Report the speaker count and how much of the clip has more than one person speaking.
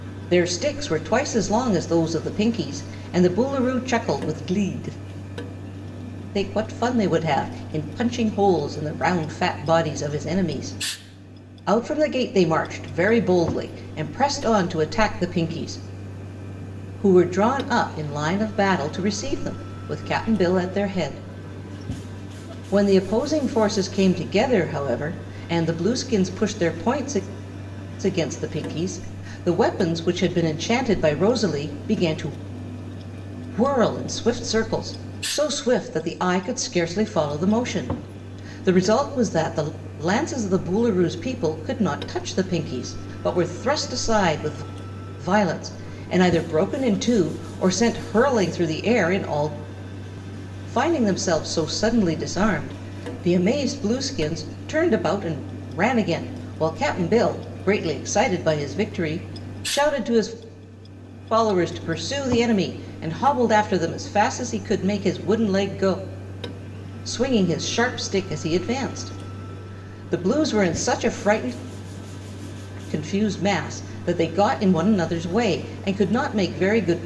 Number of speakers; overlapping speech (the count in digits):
1, no overlap